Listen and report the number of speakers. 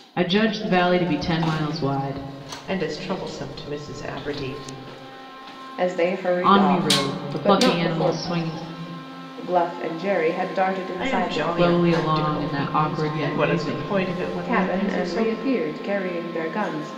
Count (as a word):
three